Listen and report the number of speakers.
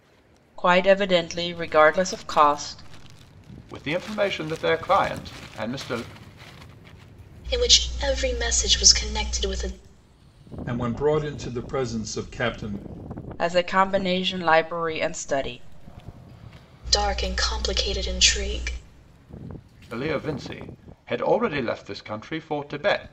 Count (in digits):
4